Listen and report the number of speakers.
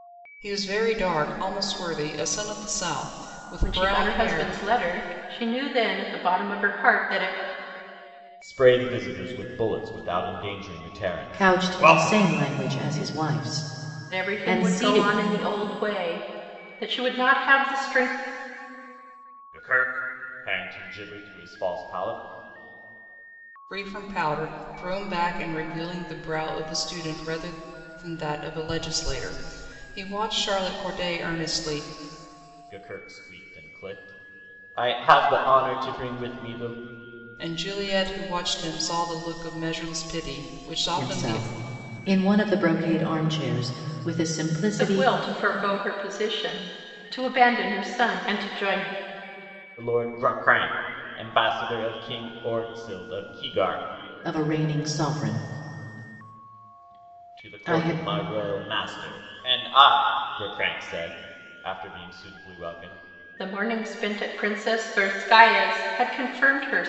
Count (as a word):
four